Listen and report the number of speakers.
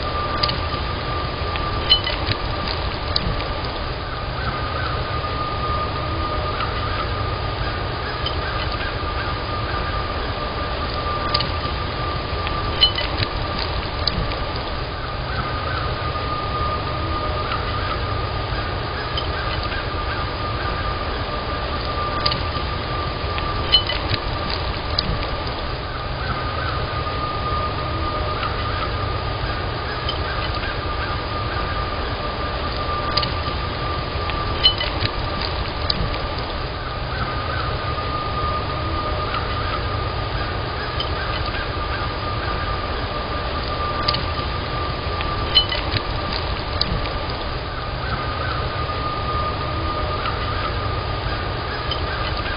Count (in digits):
0